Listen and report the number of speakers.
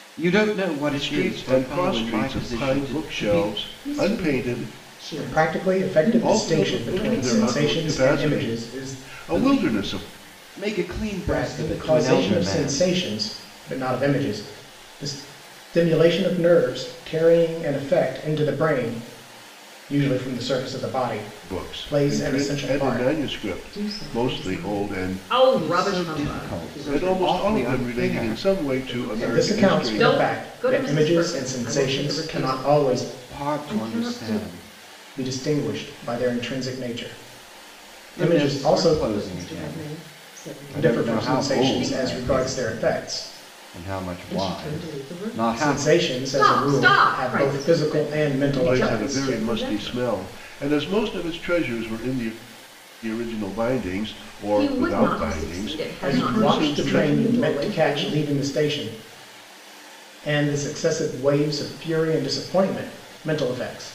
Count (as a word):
four